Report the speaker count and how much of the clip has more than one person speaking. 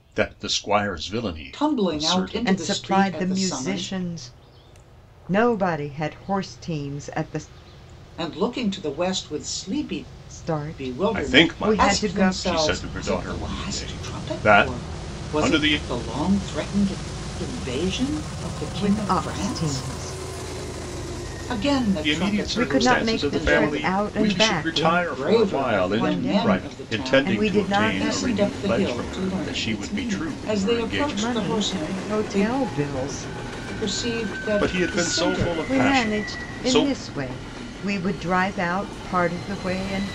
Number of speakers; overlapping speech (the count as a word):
three, about 54%